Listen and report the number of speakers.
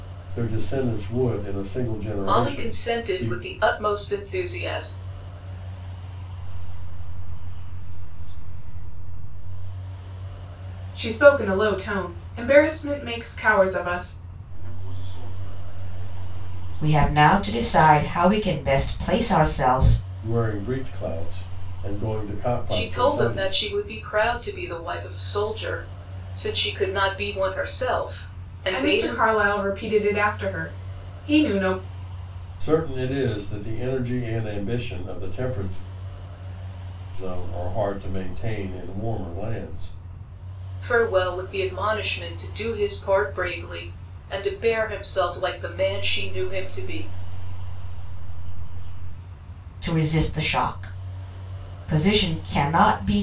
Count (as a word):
six